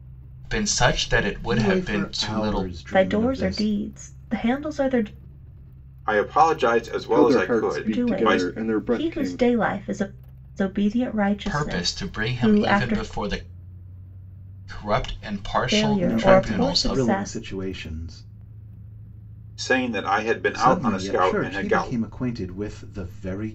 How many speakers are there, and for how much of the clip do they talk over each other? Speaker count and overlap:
5, about 40%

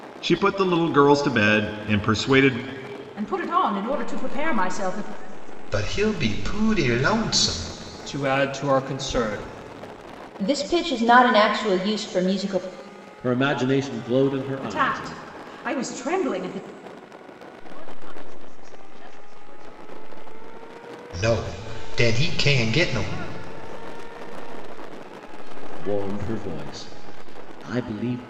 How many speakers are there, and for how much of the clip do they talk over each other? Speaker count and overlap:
7, about 17%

